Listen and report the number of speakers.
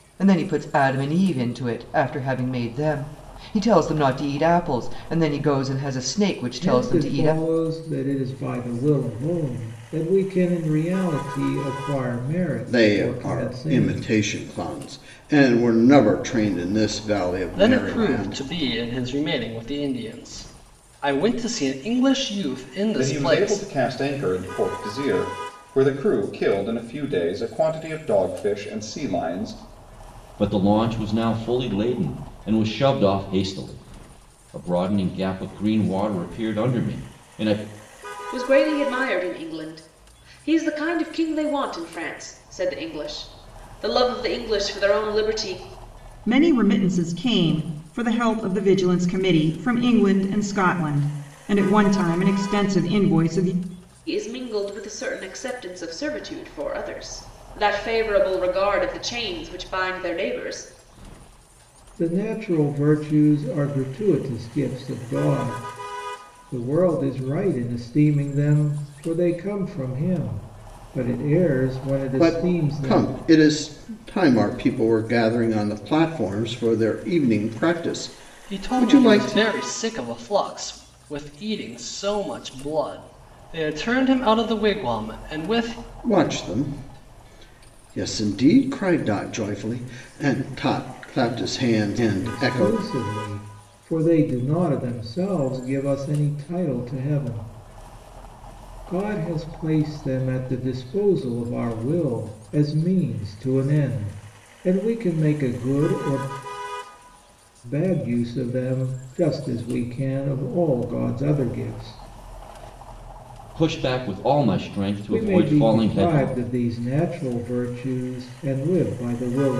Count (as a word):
eight